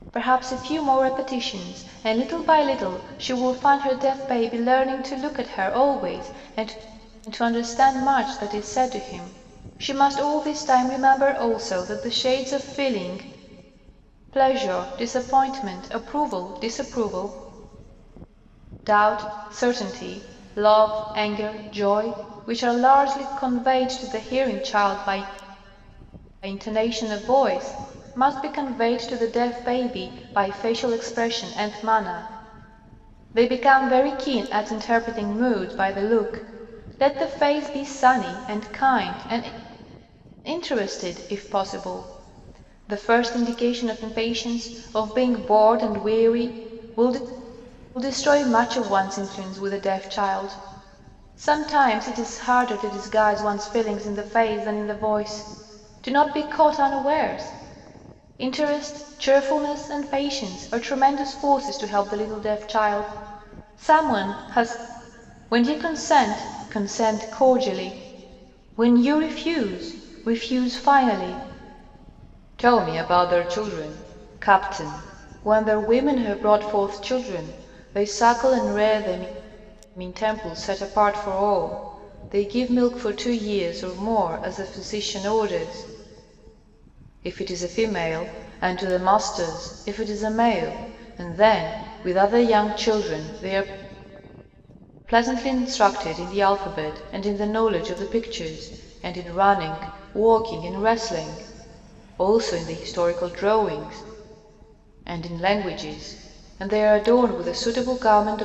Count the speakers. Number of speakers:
one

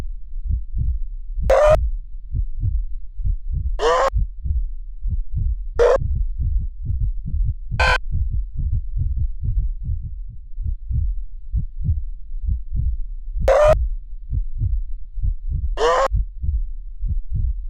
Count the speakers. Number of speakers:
zero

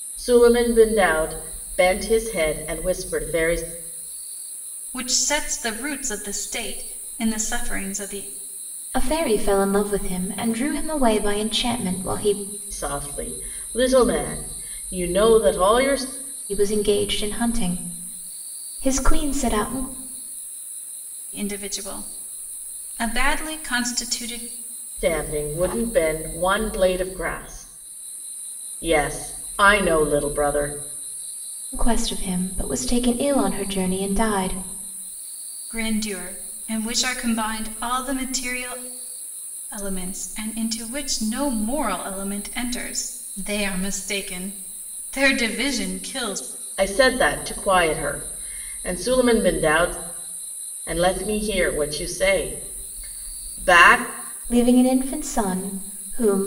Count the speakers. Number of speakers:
three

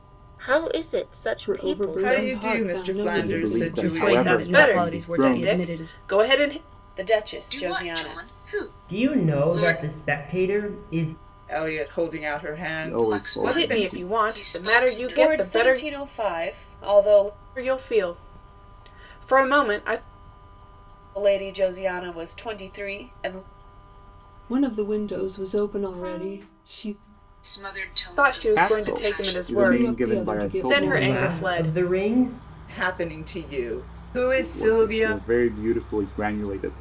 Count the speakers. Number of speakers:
nine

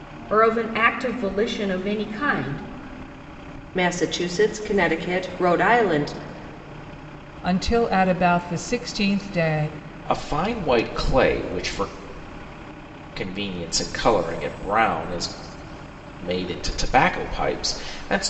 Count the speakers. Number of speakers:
four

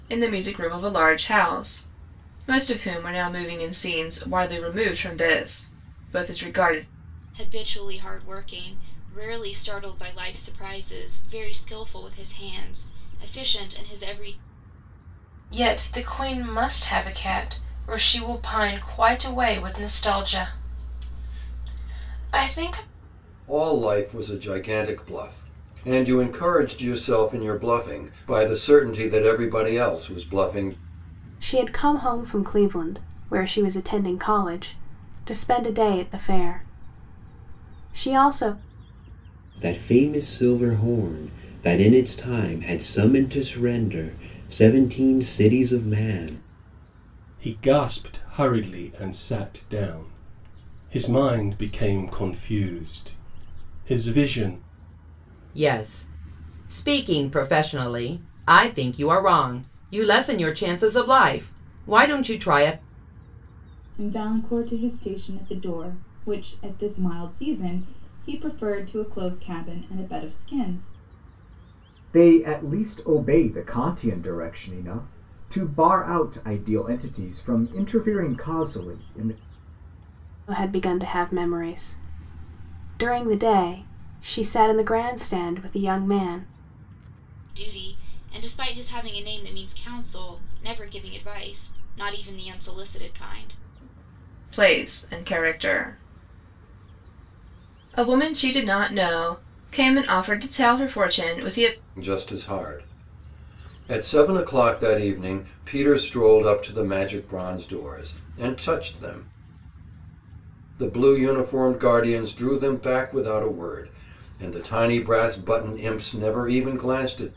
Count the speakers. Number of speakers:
ten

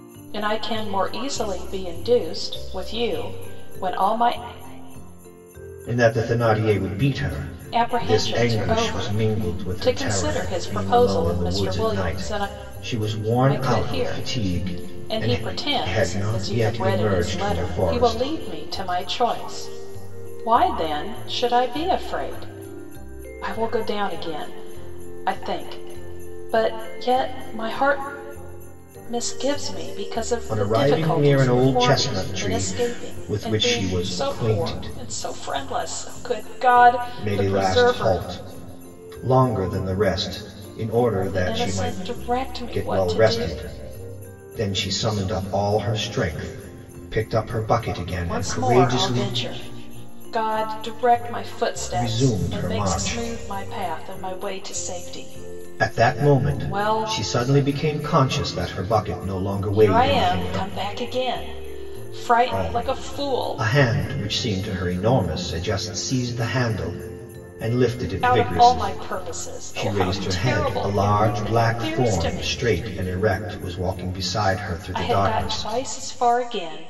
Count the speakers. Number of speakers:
two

